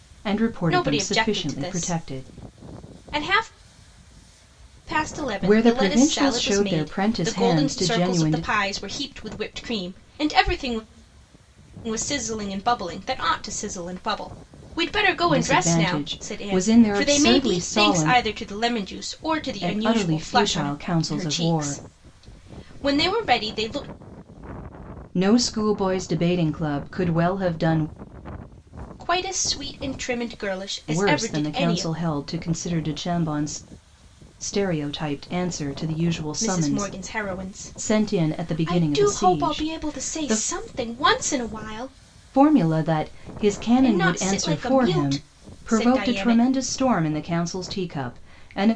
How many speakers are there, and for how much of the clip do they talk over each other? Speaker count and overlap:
2, about 33%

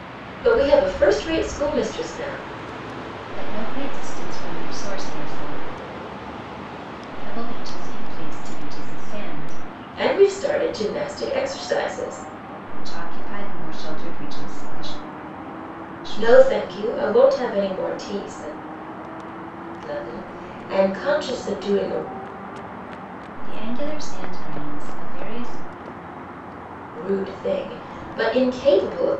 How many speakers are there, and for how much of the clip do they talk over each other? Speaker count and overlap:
2, about 1%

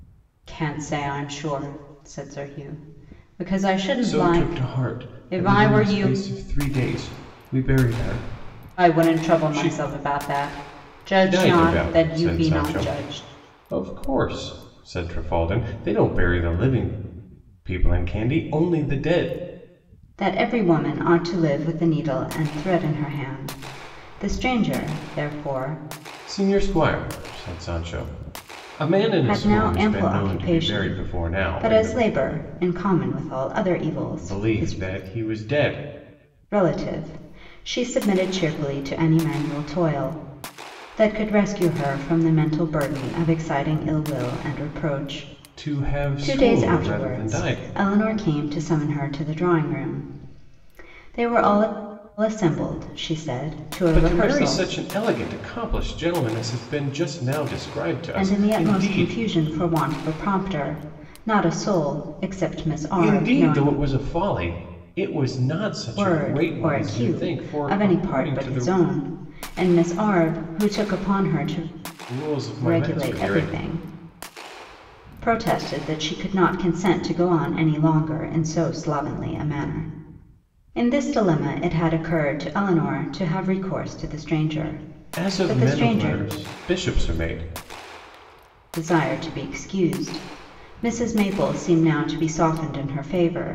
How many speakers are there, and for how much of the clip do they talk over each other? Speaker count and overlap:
2, about 19%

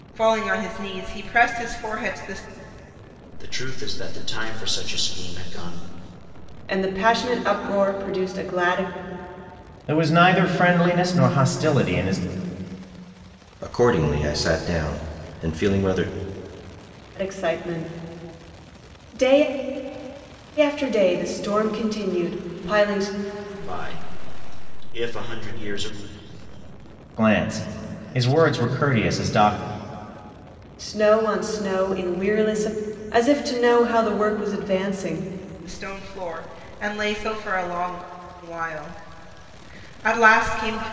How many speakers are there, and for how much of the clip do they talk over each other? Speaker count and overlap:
5, no overlap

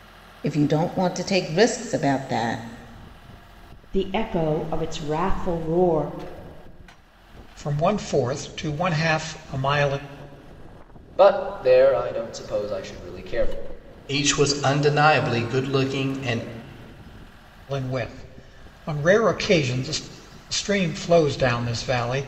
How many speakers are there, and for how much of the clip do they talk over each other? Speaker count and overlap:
5, no overlap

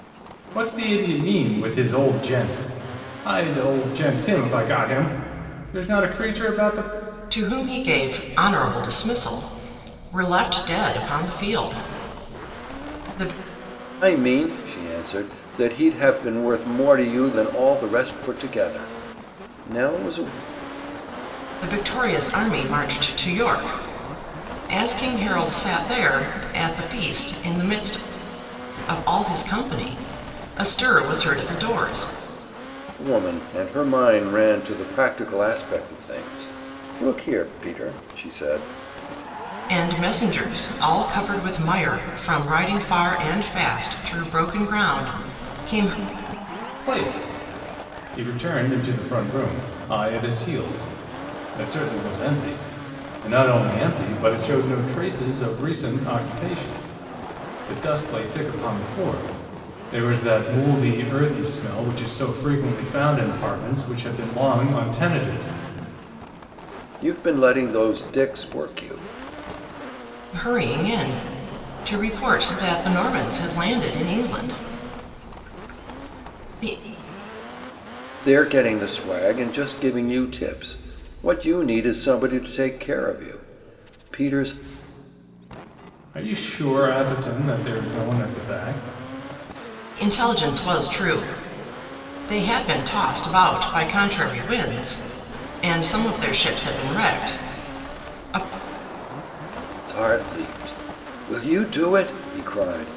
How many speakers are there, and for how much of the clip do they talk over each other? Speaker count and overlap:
3, no overlap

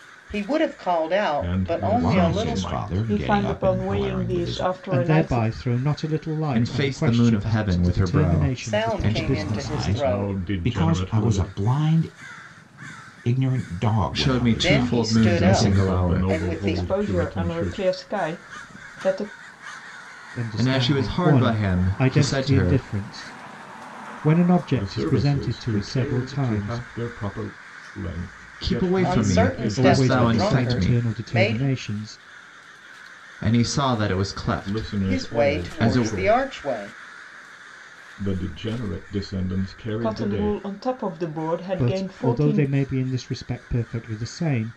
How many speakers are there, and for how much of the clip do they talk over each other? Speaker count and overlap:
6, about 53%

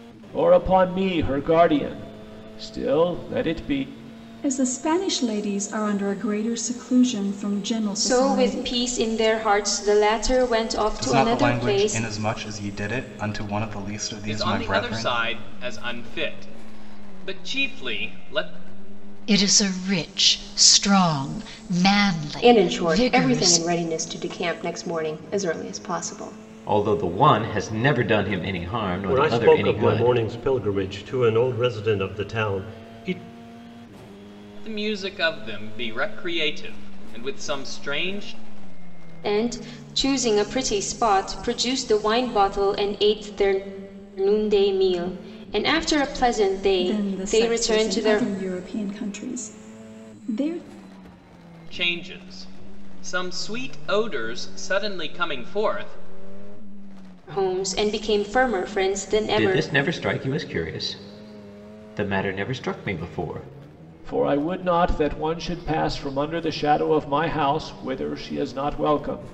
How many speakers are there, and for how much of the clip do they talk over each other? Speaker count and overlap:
9, about 10%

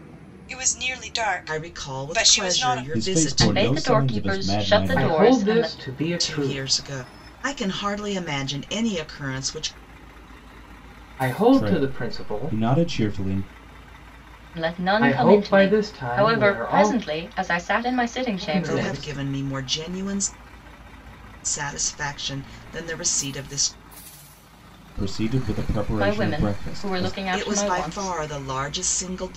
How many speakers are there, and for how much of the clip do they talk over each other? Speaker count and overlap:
5, about 37%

